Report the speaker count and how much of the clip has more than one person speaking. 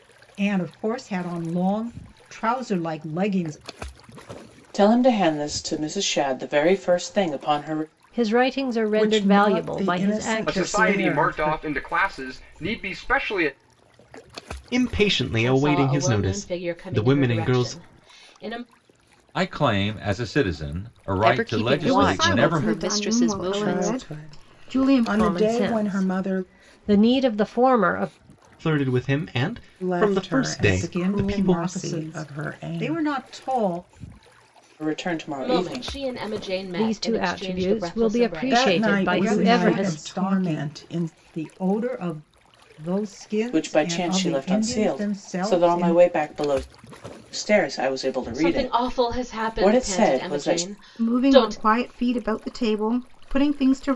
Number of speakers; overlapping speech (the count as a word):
ten, about 45%